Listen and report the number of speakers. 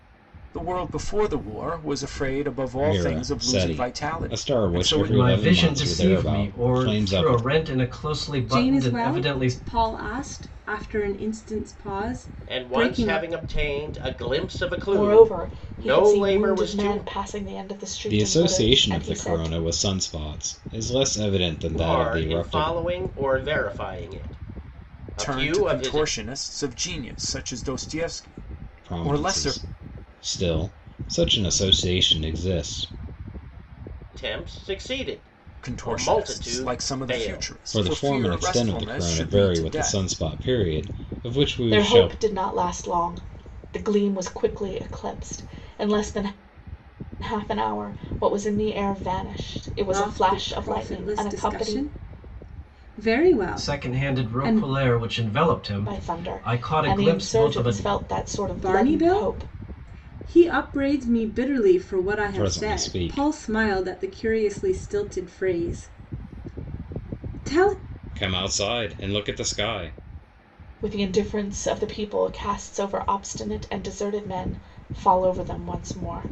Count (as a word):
six